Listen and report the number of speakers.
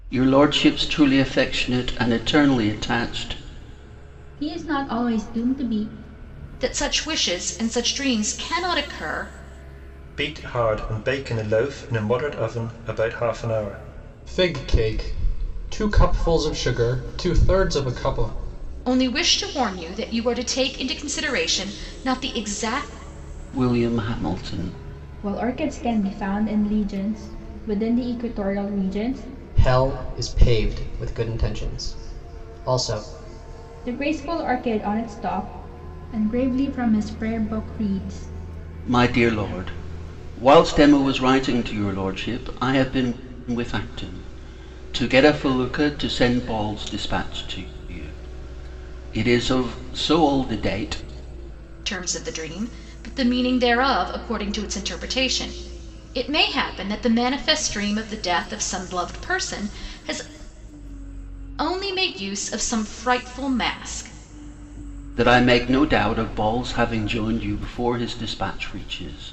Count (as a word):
four